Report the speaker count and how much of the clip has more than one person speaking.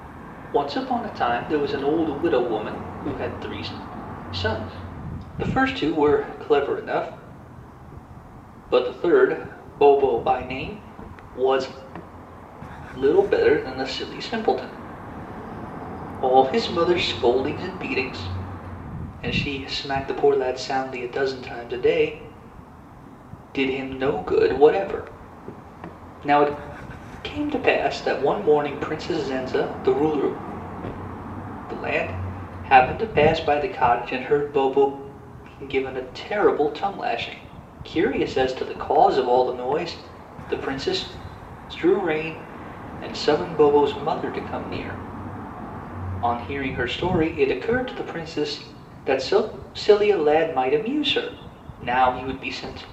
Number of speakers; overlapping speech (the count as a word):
one, no overlap